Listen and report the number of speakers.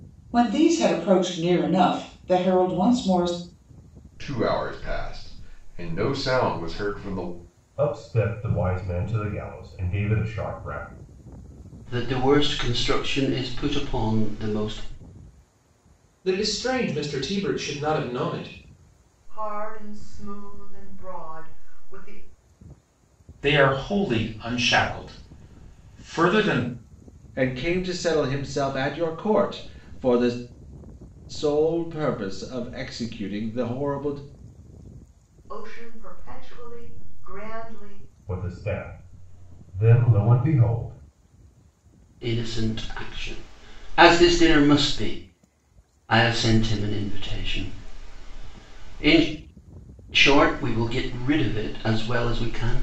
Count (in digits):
8